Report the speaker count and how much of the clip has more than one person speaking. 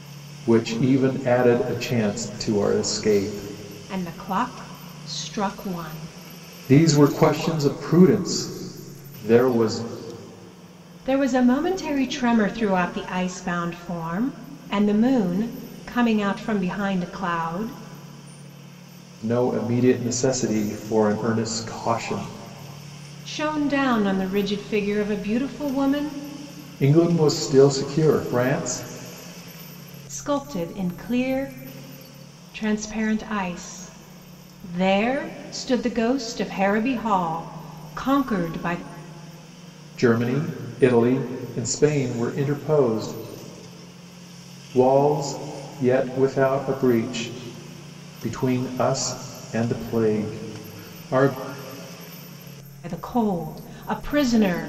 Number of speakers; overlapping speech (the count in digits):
2, no overlap